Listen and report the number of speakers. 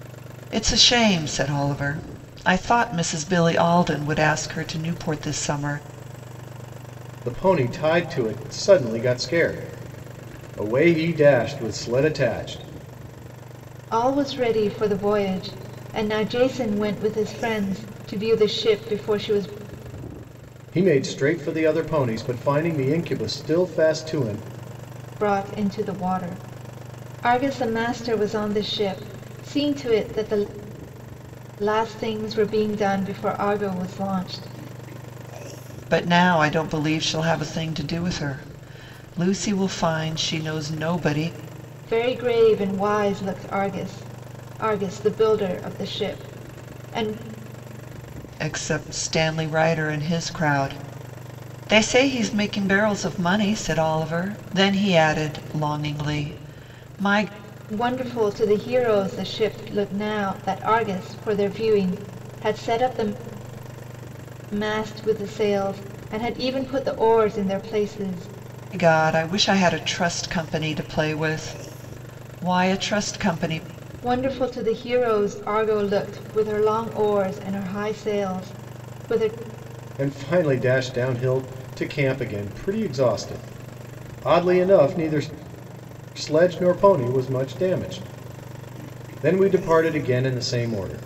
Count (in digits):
3